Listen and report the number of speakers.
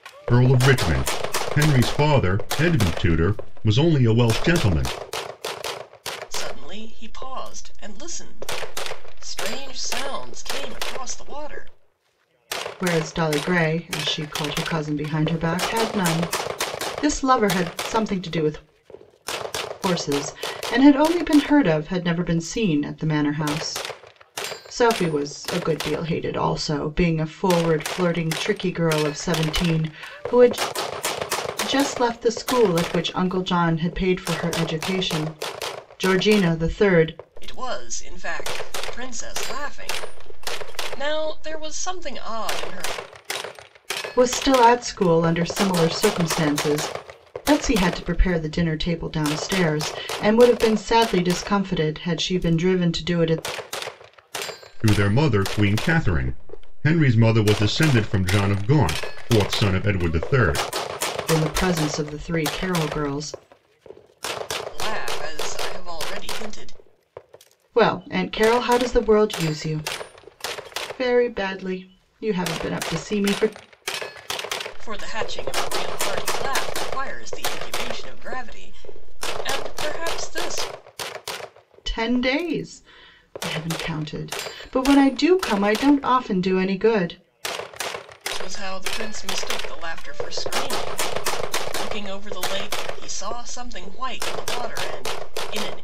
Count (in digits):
3